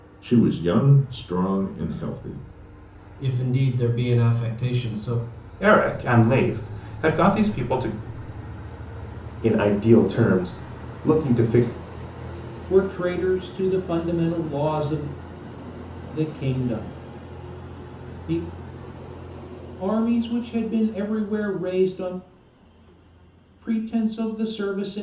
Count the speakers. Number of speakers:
5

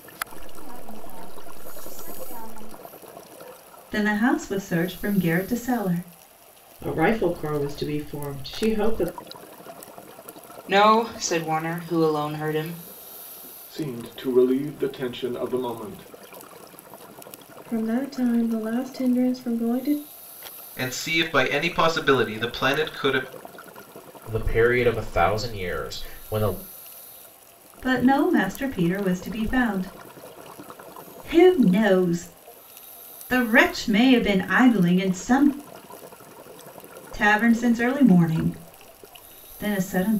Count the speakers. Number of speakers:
8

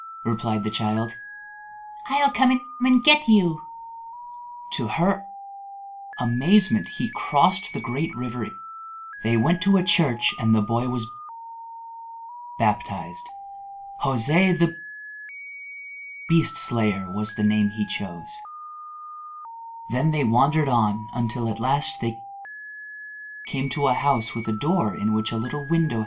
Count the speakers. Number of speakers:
1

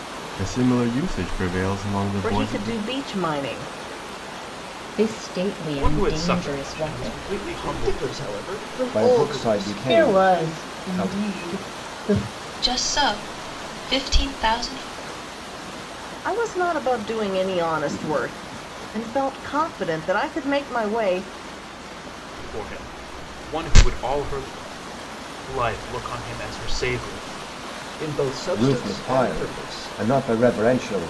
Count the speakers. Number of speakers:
8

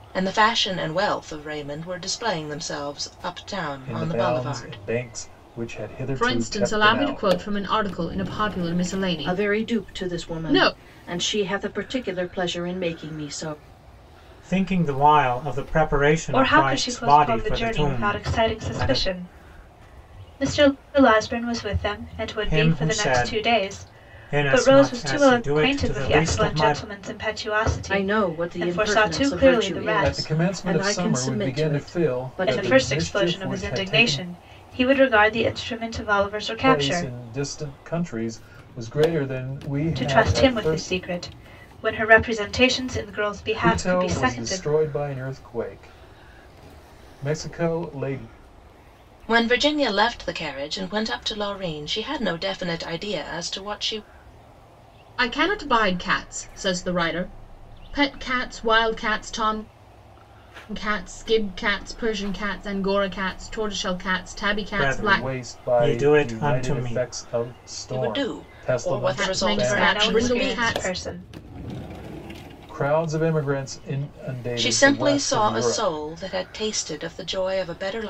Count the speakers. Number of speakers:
6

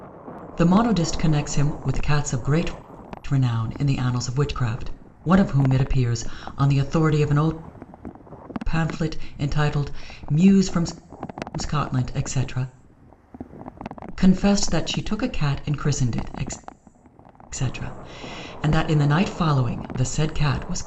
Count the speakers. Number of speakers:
1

